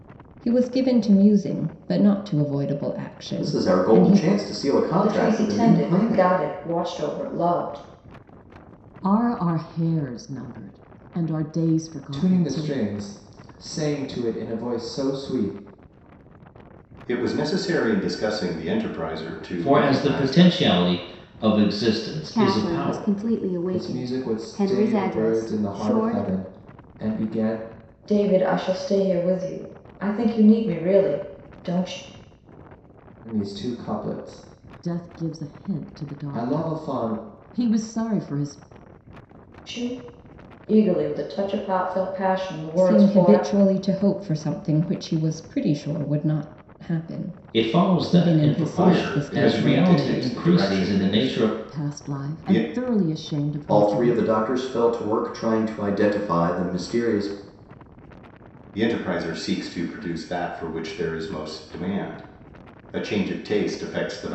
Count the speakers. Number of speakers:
eight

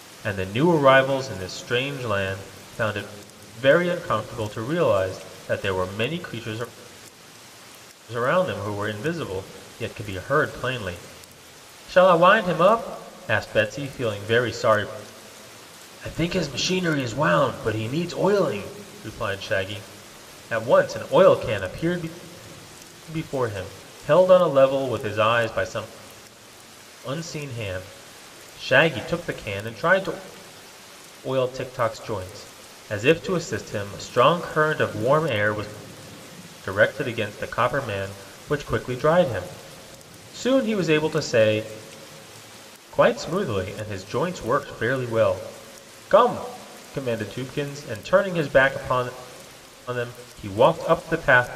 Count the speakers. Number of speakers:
one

